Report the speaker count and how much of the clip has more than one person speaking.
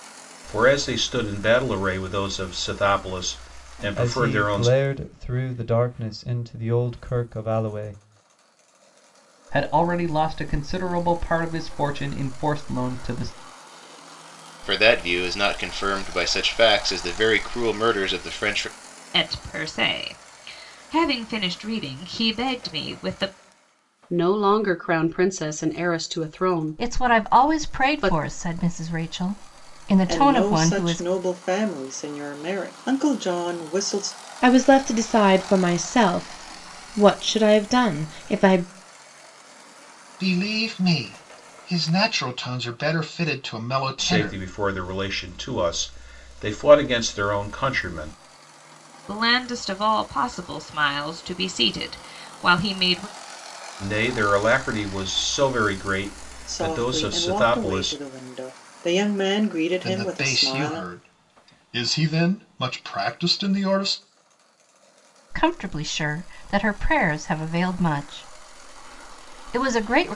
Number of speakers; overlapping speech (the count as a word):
ten, about 9%